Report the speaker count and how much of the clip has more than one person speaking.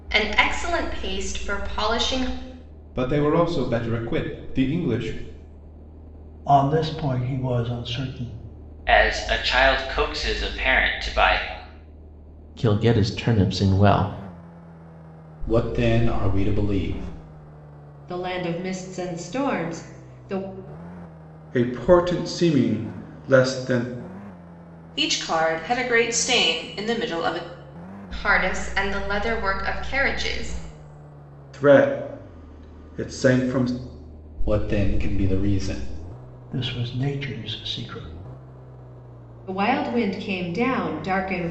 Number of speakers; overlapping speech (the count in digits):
9, no overlap